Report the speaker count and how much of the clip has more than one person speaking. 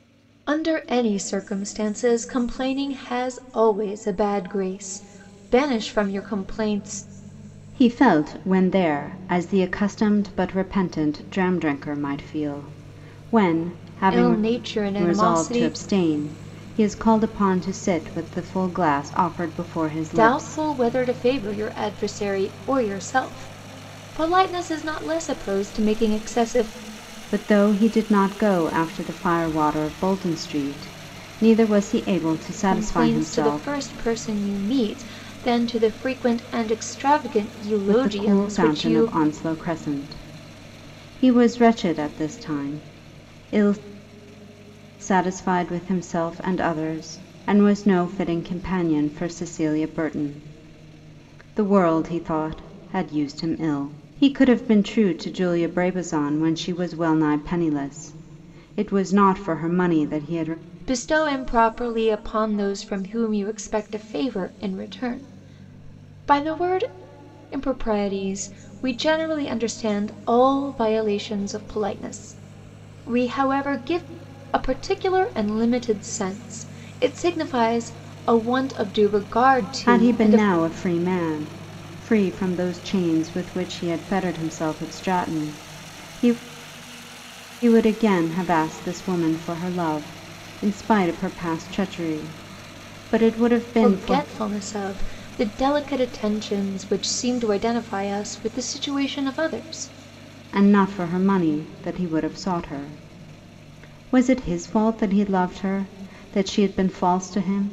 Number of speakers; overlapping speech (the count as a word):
two, about 5%